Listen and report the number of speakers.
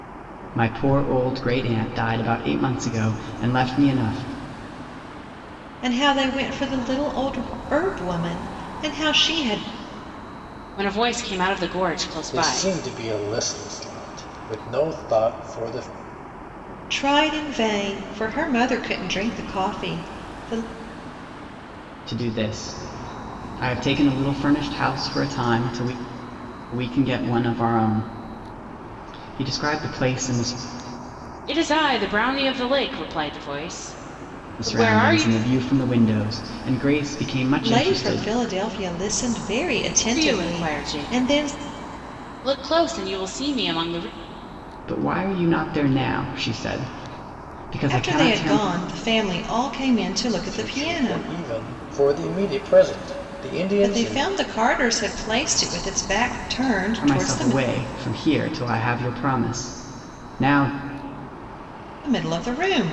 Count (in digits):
4